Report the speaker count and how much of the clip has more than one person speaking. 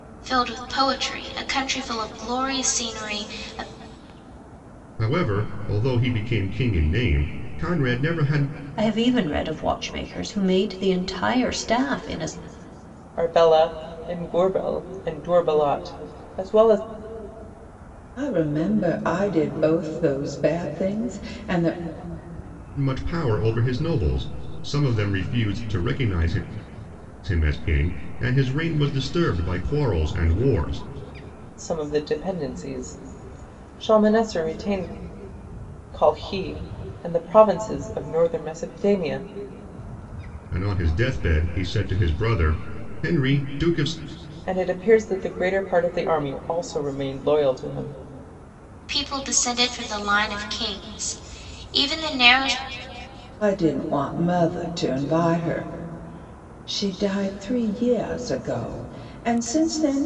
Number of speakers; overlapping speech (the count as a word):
five, no overlap